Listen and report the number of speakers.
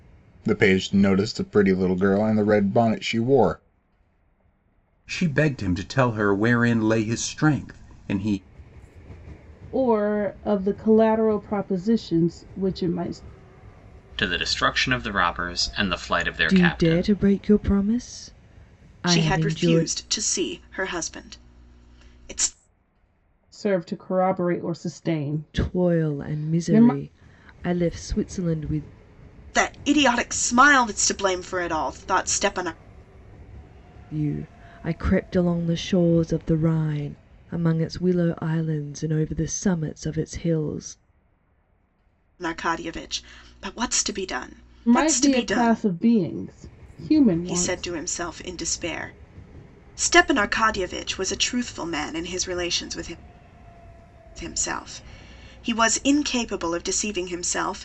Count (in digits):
6